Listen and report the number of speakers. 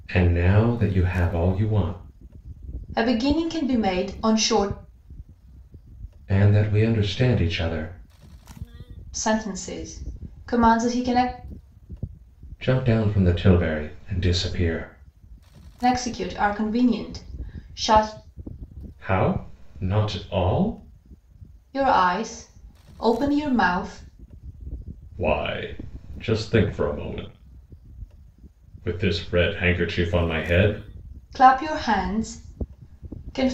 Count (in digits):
2